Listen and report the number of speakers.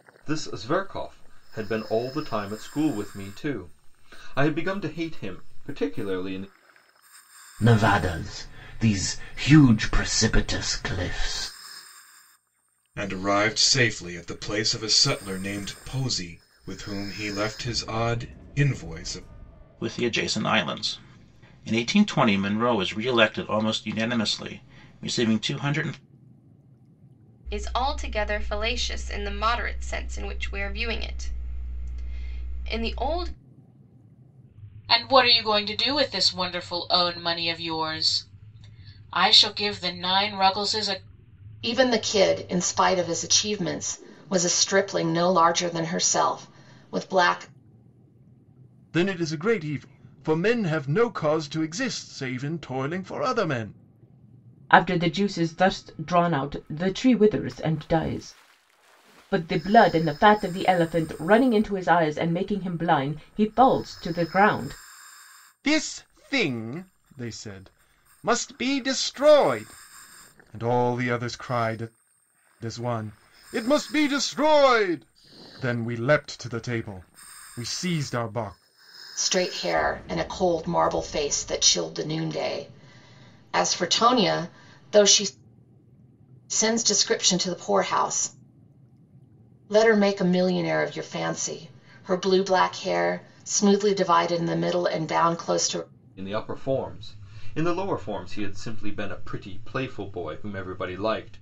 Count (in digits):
9